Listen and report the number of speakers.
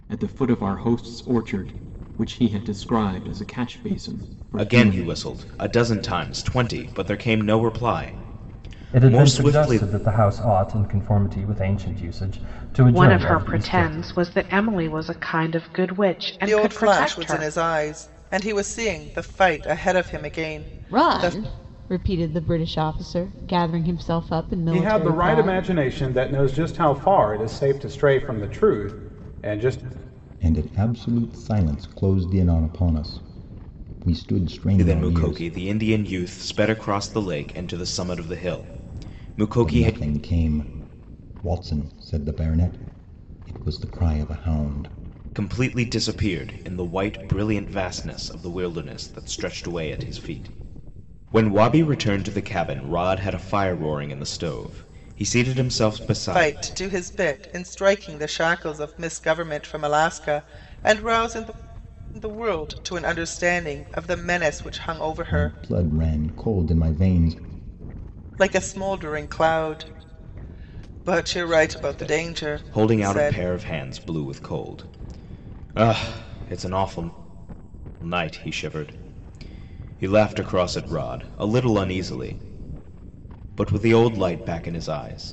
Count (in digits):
8